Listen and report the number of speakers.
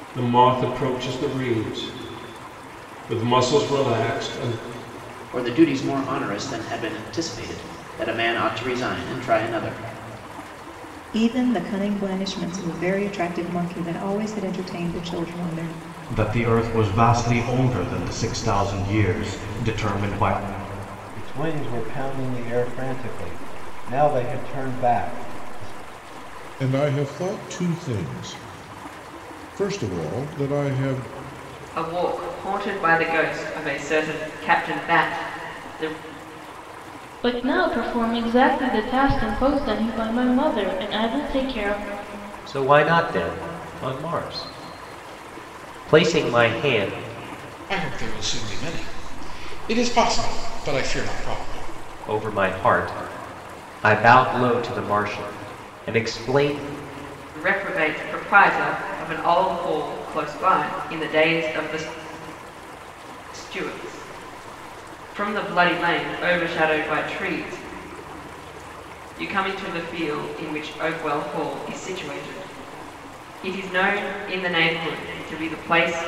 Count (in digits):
10